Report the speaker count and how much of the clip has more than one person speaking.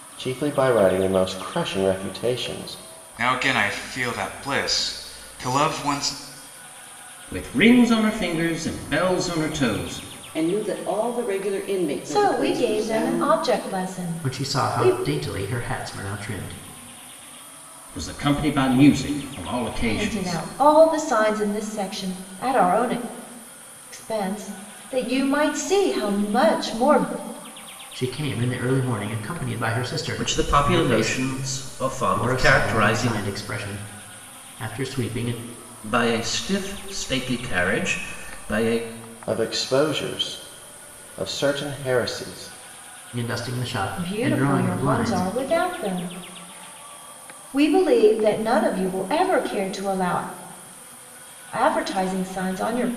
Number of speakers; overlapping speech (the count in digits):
6, about 12%